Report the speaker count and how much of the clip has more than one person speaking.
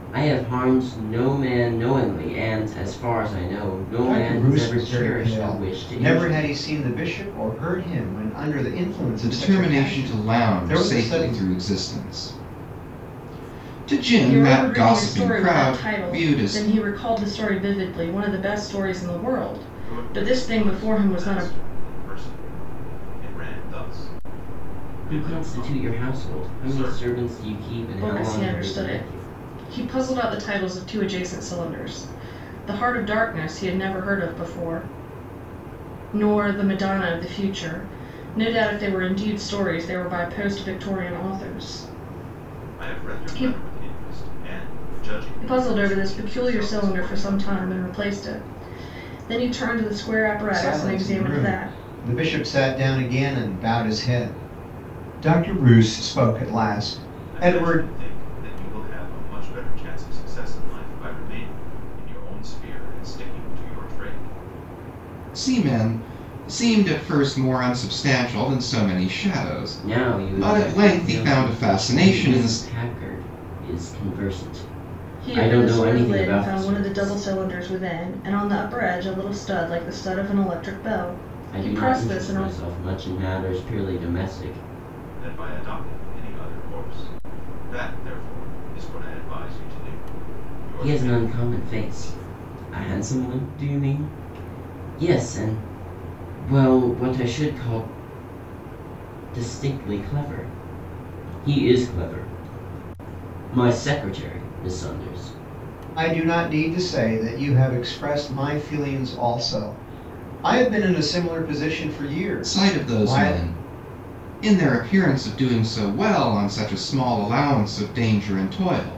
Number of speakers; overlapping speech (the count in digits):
5, about 21%